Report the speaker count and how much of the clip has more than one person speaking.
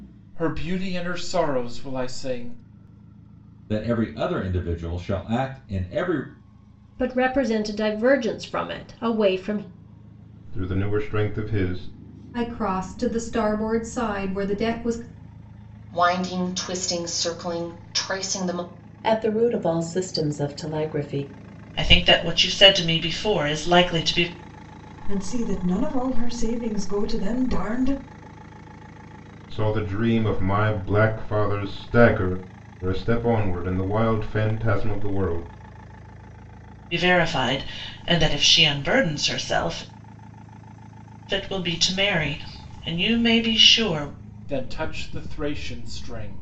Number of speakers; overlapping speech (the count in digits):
9, no overlap